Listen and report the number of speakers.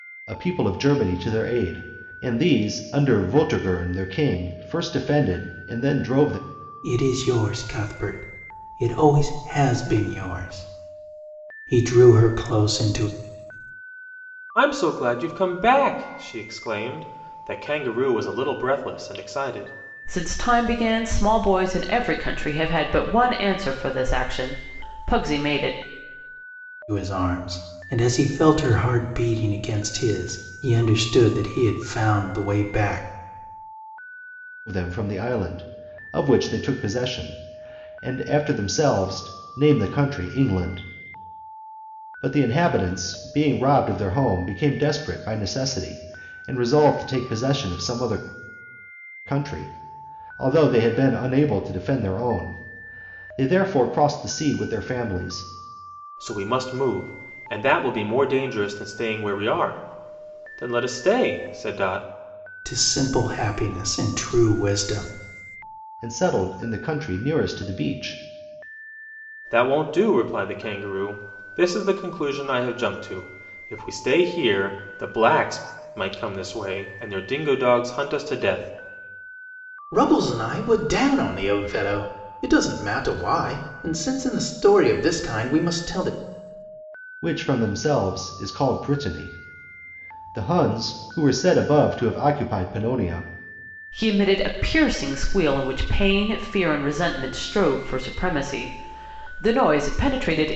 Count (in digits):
4